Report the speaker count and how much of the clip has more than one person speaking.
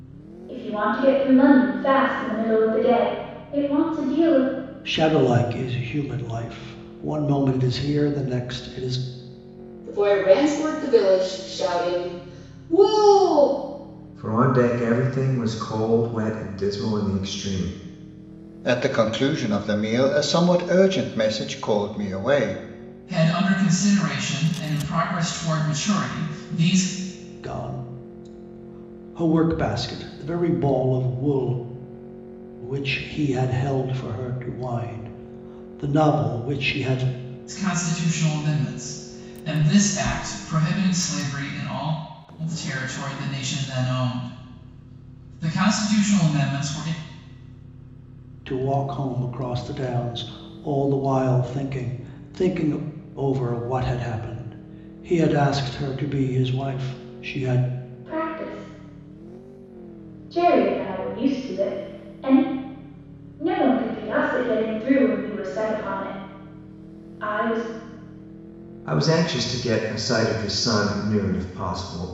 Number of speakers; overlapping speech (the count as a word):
six, no overlap